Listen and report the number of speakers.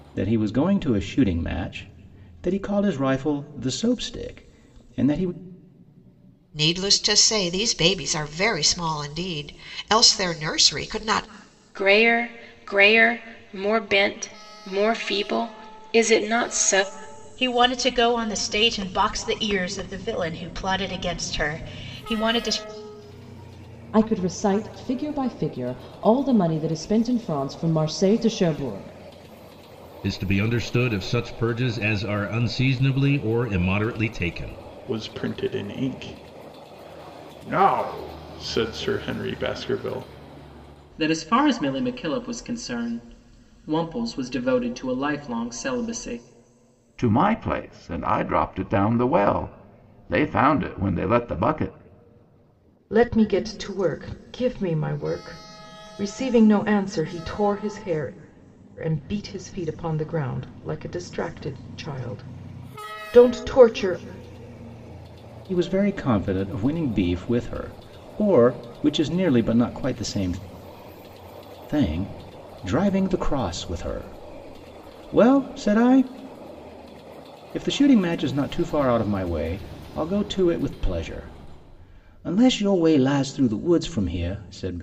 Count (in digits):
10